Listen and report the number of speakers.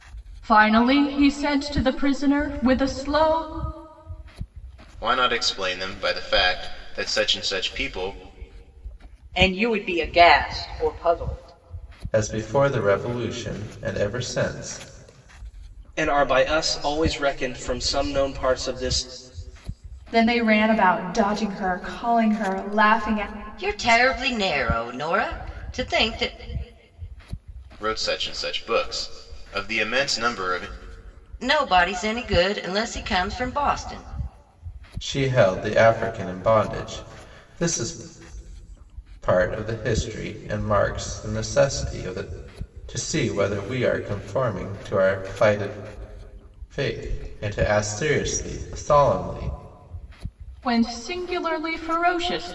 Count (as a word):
seven